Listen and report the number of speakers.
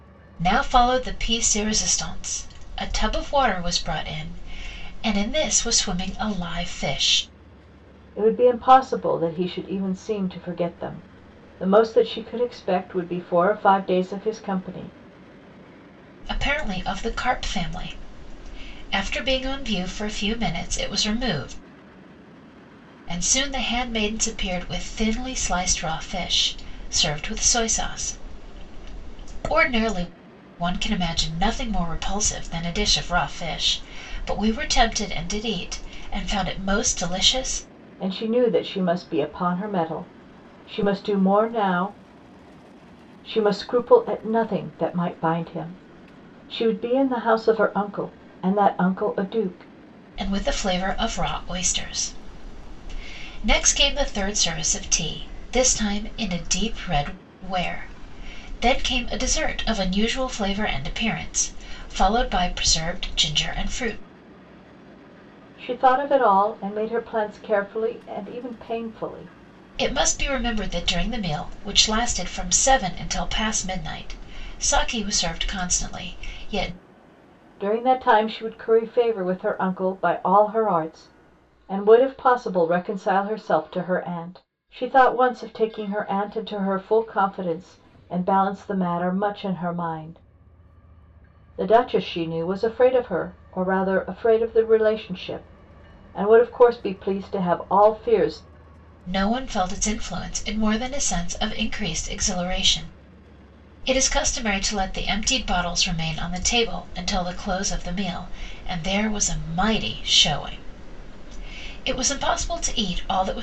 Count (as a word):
two